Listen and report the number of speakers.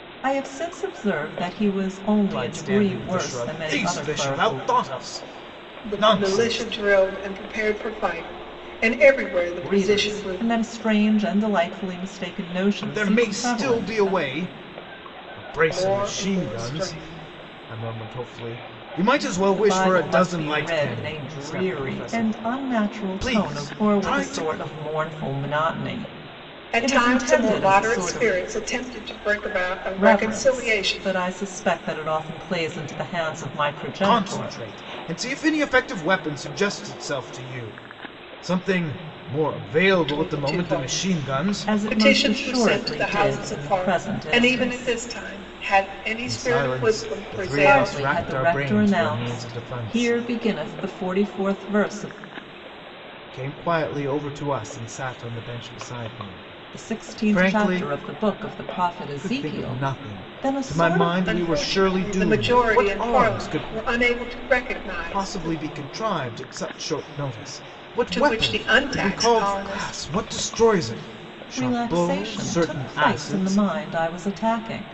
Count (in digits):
3